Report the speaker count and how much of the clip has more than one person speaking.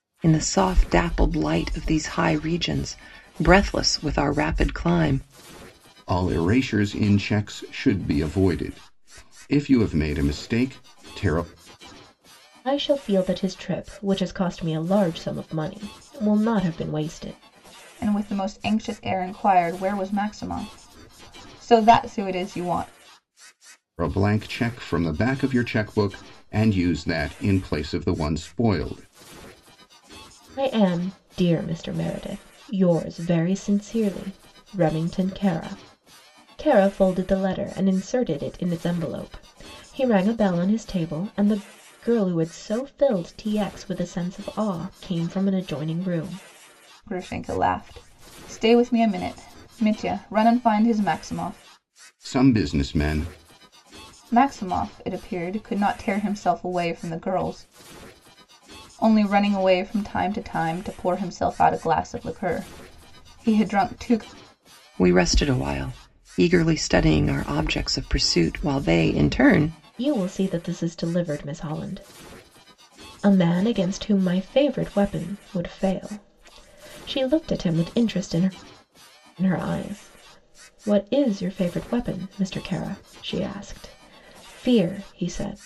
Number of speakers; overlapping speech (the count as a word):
four, no overlap